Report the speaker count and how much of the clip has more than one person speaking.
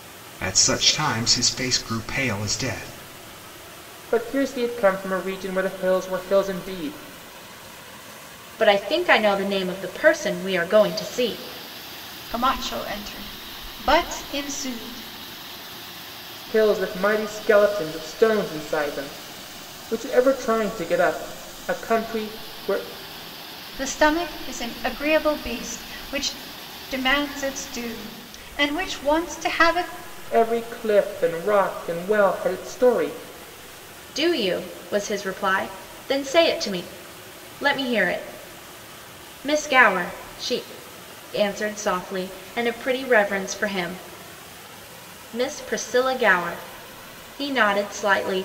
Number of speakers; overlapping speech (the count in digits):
4, no overlap